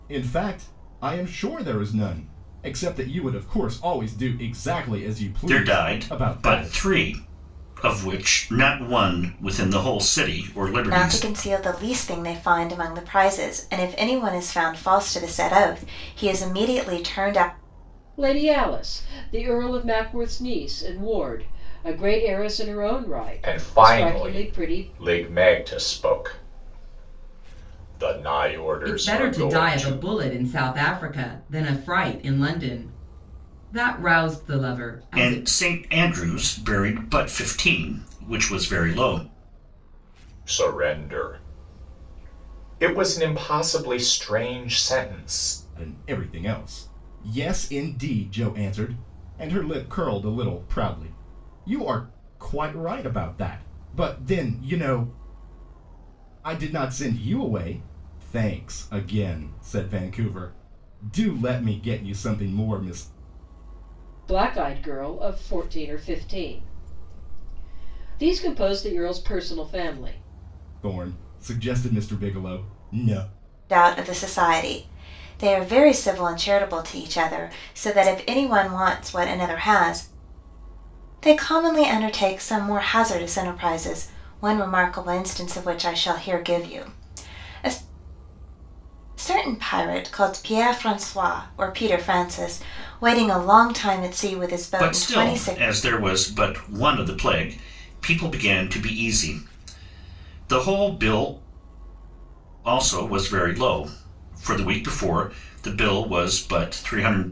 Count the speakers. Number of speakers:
6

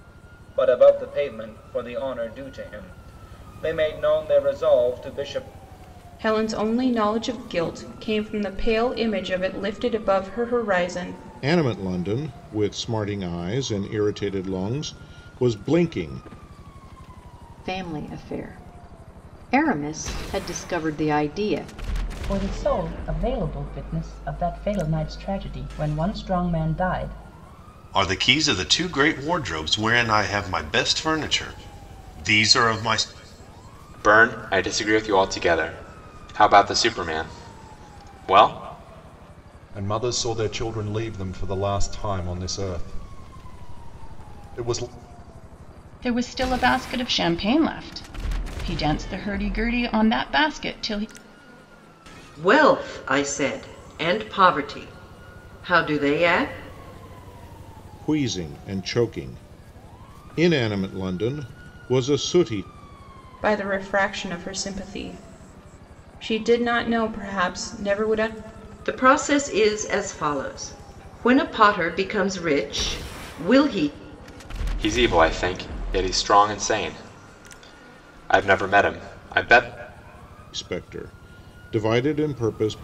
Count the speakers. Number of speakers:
10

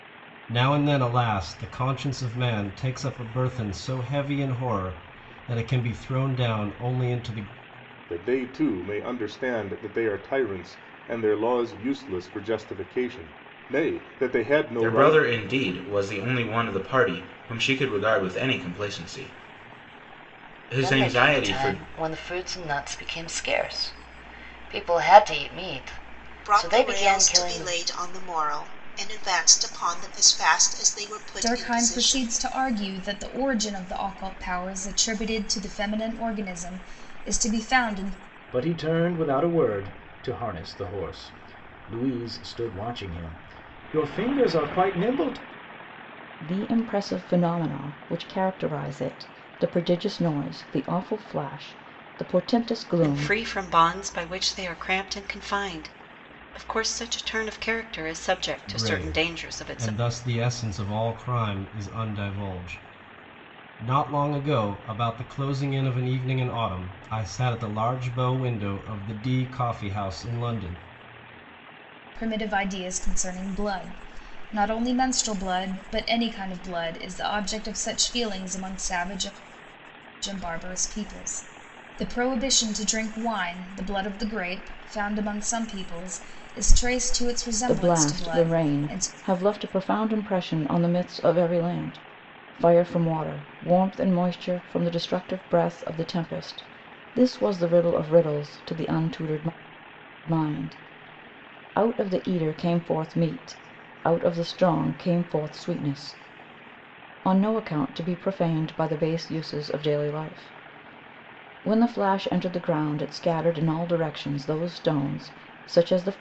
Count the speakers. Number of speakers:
9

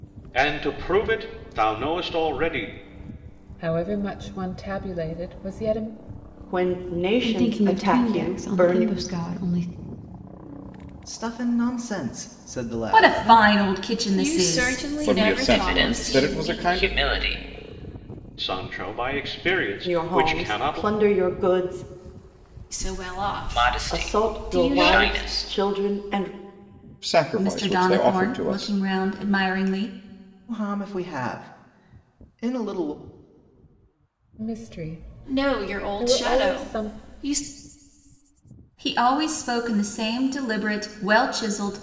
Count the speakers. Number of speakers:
9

